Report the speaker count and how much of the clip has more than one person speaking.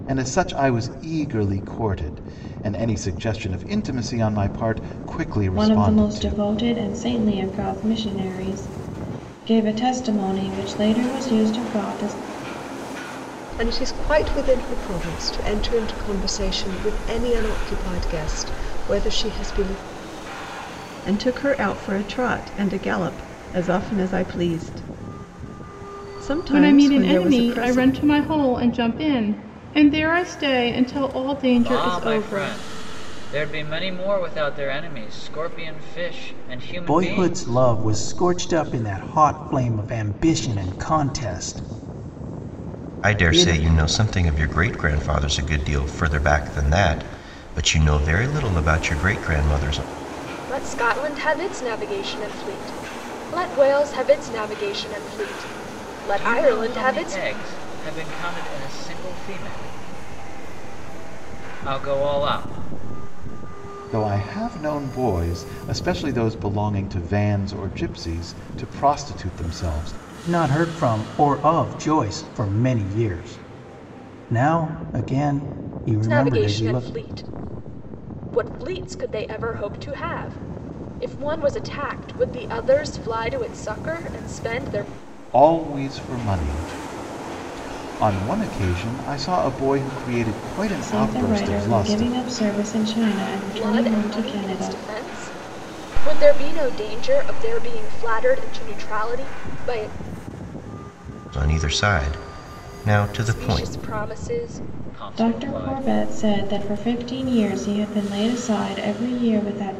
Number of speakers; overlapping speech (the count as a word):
nine, about 10%